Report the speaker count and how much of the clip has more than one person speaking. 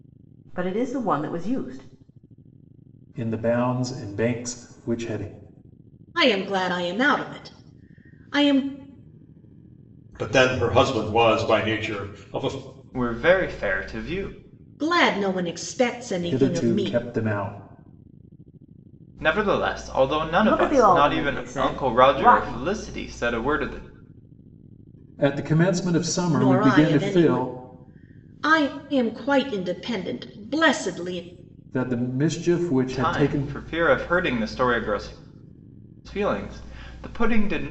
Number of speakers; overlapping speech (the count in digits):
5, about 12%